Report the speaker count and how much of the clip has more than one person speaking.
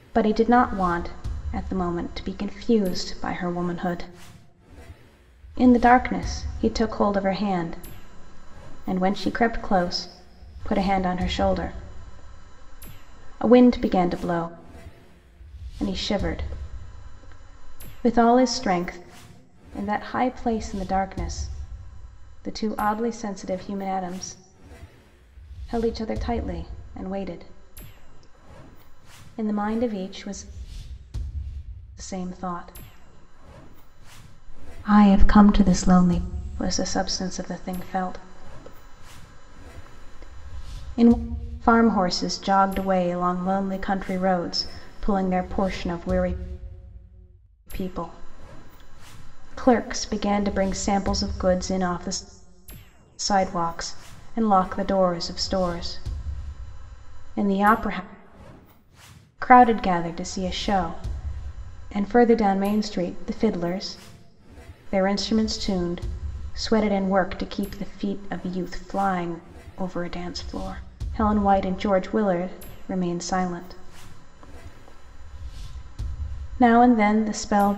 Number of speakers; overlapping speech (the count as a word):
one, no overlap